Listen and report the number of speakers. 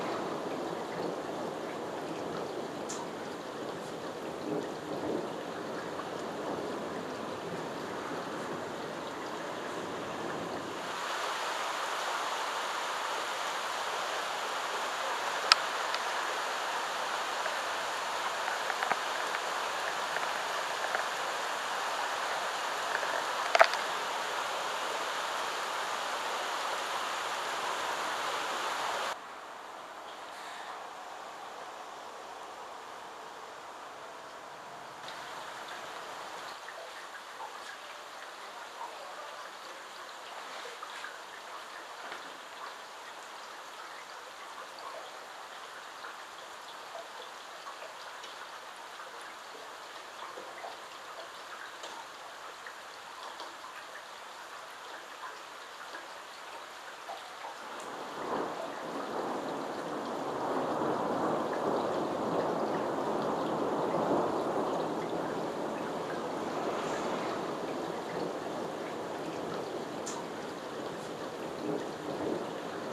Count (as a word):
zero